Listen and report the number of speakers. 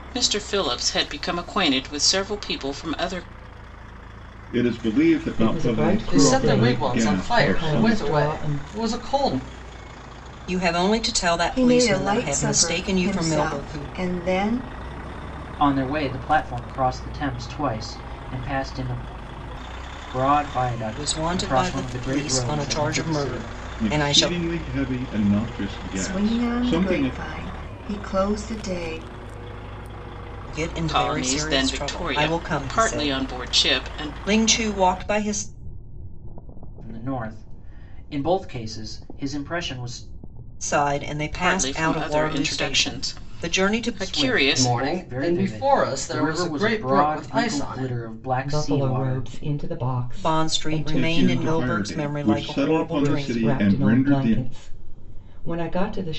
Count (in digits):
7